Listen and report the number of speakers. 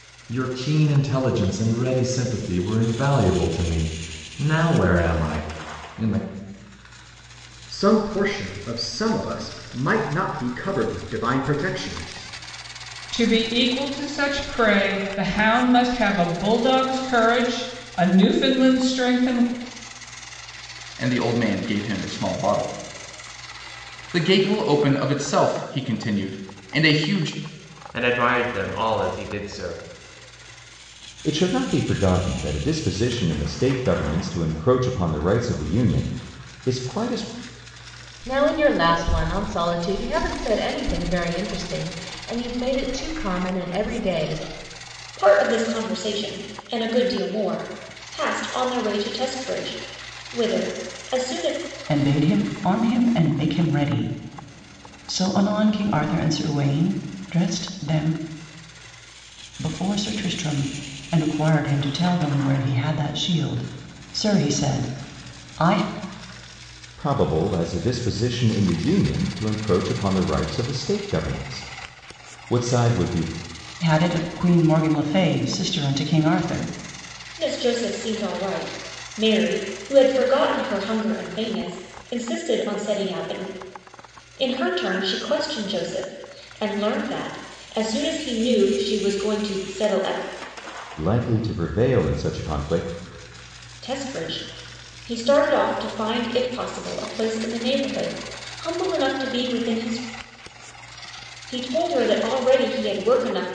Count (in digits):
9